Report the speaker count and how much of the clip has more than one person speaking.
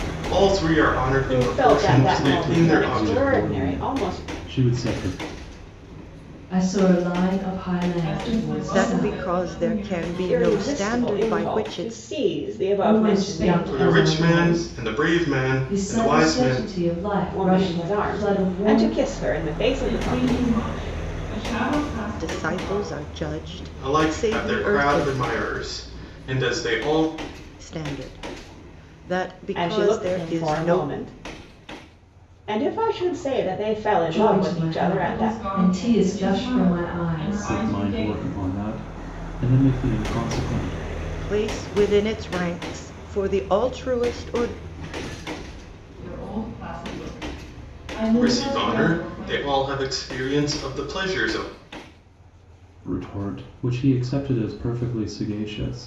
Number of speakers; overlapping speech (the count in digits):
6, about 38%